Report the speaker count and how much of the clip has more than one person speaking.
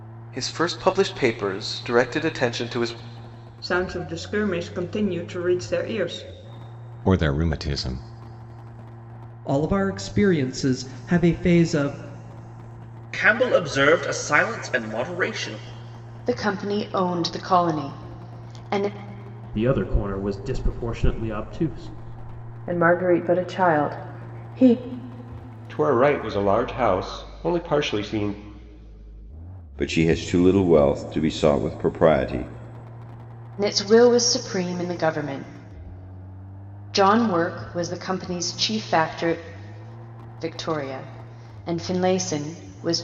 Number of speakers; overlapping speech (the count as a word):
ten, no overlap